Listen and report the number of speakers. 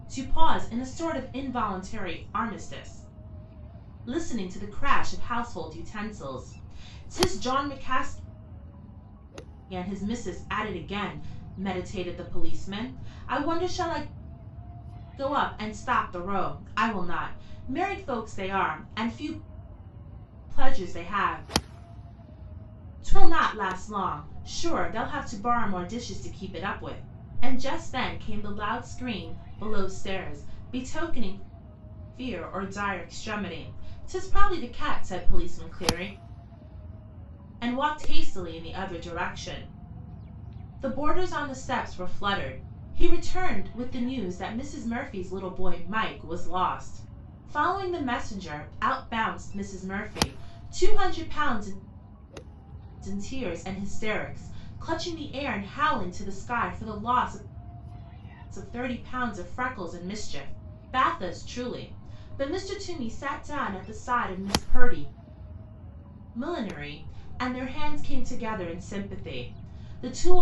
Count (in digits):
1